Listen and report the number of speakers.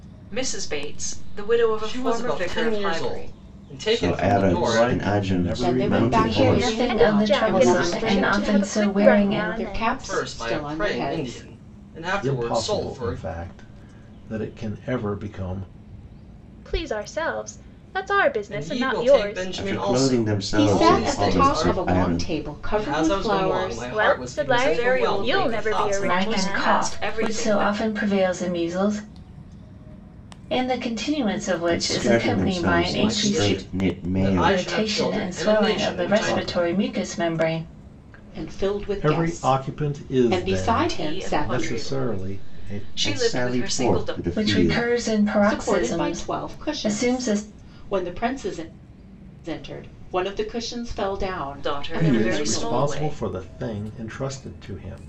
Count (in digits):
7